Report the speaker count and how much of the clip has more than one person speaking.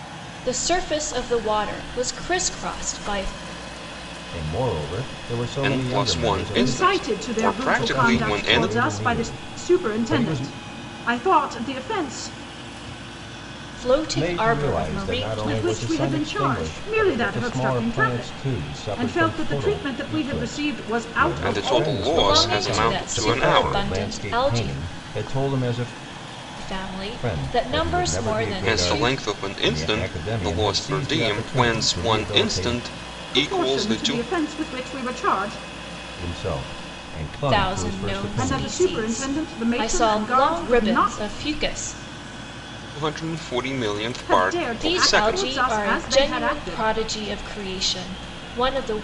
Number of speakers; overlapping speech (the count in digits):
4, about 56%